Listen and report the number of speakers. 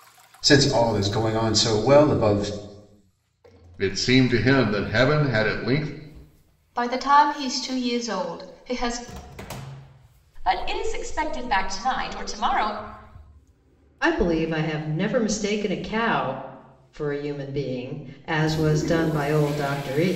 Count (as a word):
five